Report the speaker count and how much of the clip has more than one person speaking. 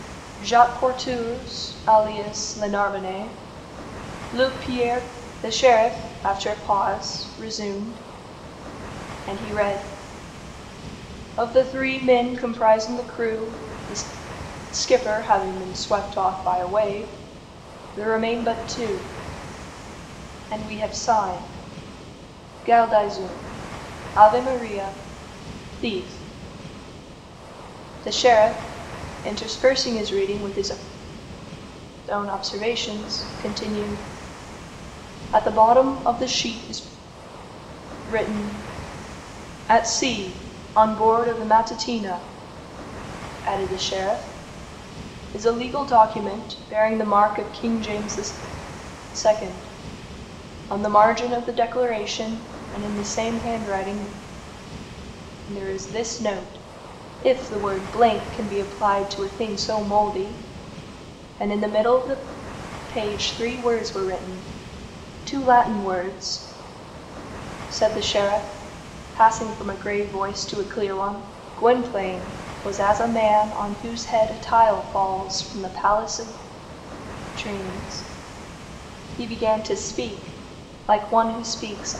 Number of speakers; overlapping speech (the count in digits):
1, no overlap